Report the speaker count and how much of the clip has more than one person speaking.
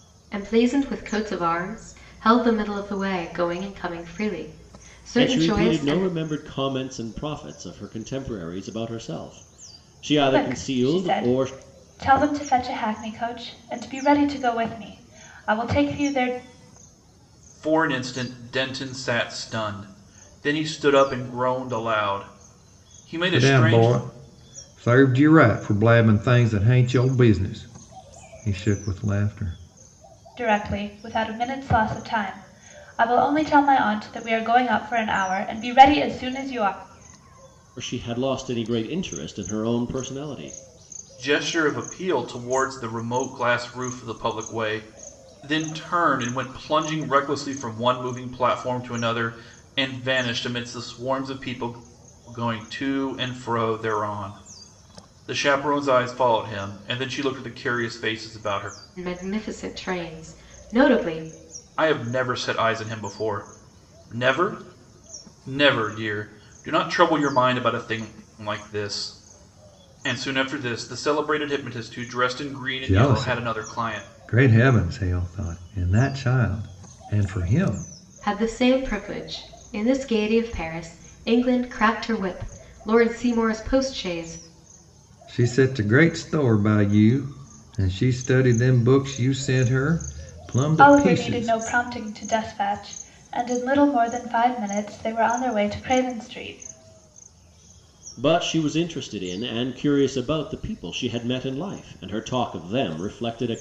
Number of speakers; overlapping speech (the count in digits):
5, about 5%